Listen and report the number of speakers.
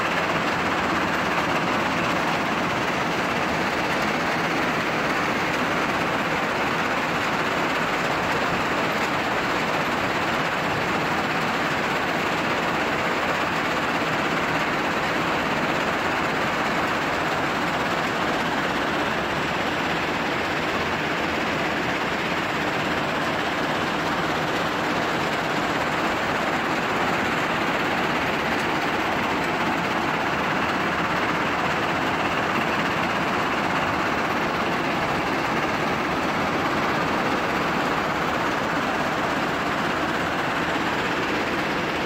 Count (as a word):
zero